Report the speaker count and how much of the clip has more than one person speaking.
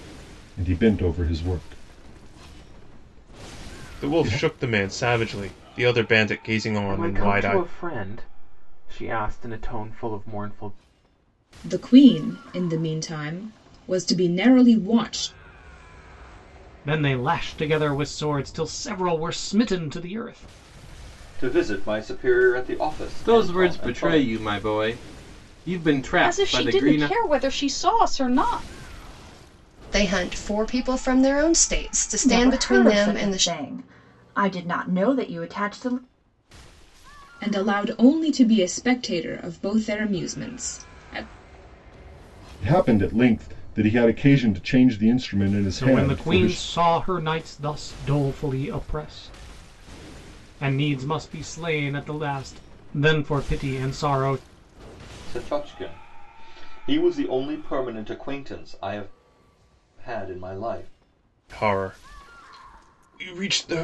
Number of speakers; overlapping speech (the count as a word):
ten, about 9%